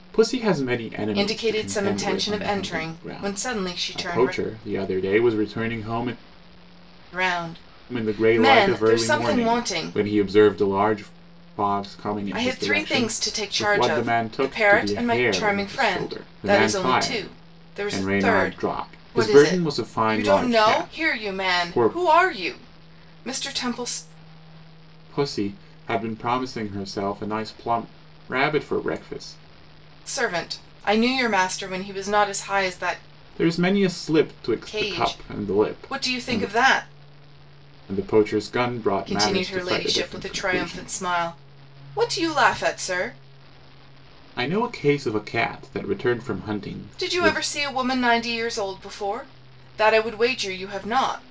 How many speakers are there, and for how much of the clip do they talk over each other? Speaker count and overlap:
two, about 38%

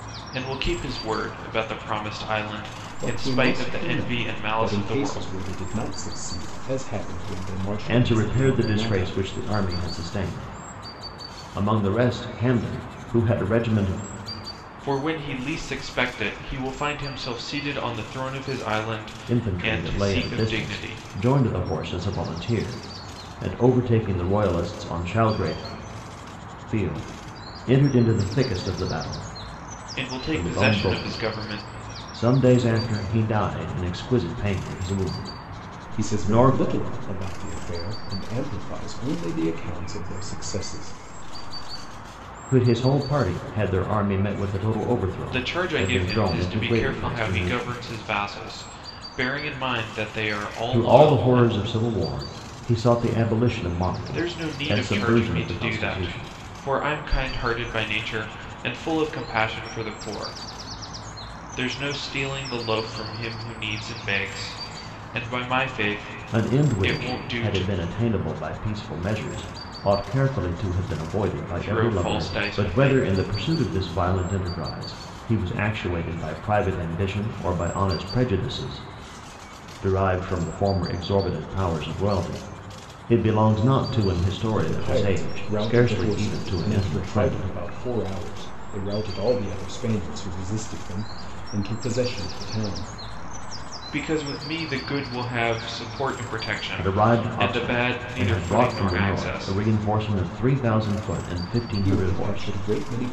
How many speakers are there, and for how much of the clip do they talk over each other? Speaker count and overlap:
three, about 22%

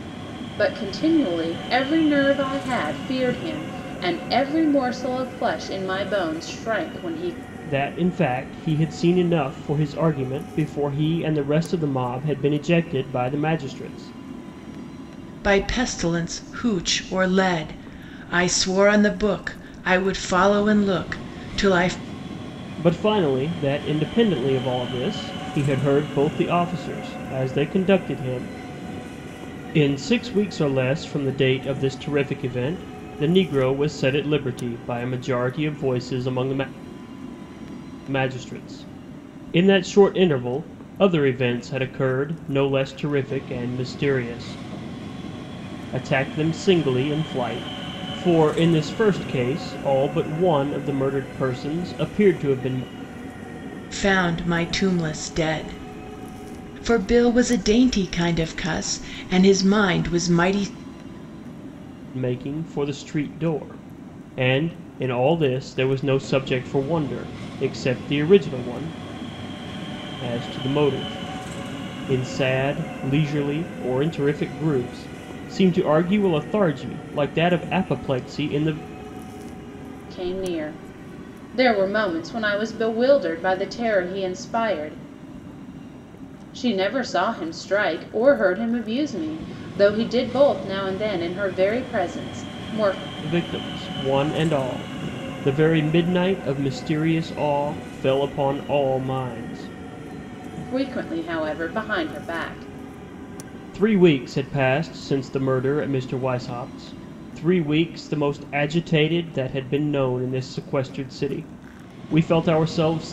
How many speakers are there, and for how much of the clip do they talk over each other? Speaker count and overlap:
three, no overlap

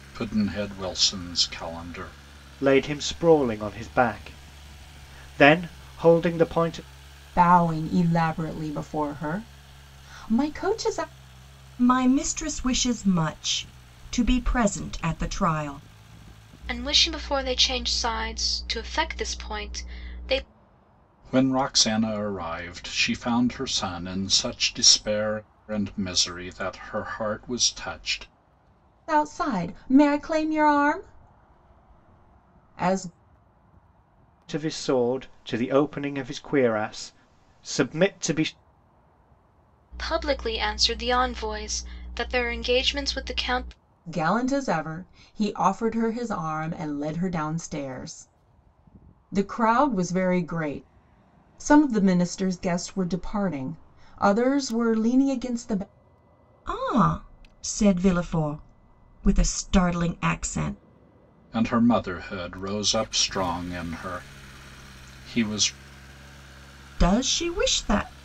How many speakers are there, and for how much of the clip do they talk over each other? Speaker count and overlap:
five, no overlap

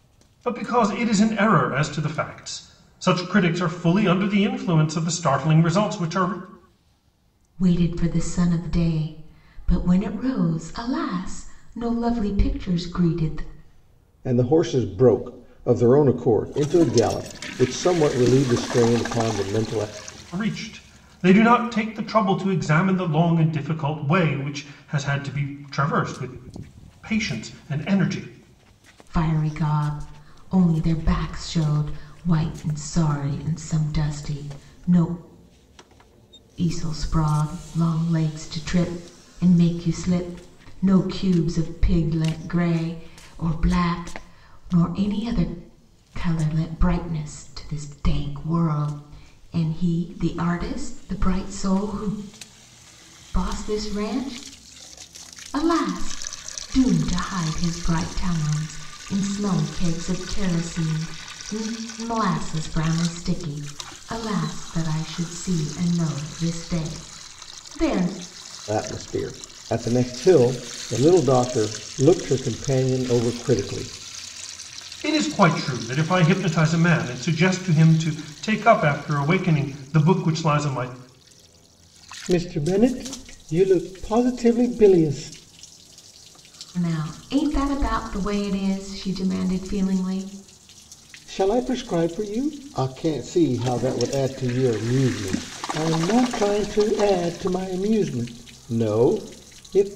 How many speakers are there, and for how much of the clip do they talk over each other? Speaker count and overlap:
three, no overlap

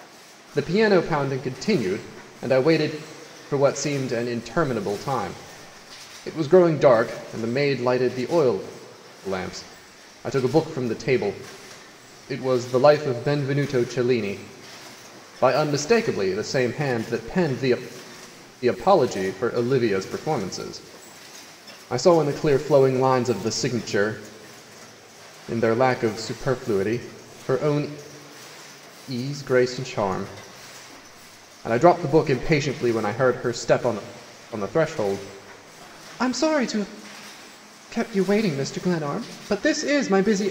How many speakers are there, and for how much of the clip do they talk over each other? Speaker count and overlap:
one, no overlap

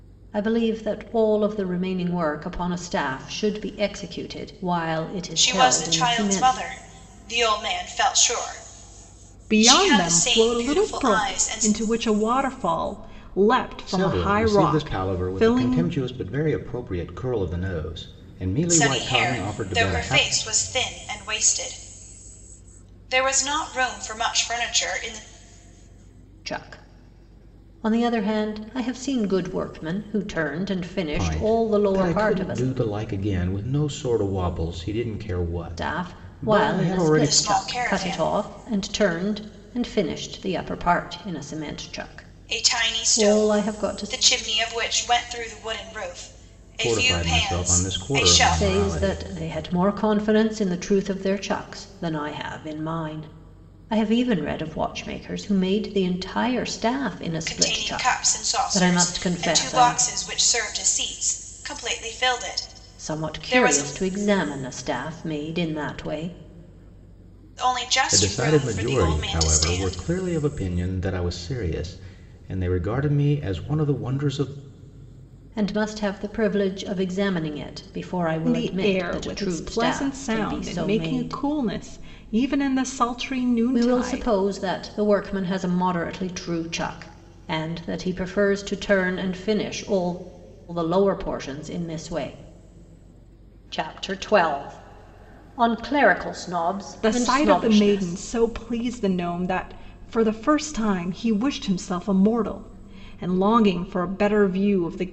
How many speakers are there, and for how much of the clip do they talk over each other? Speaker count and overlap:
four, about 25%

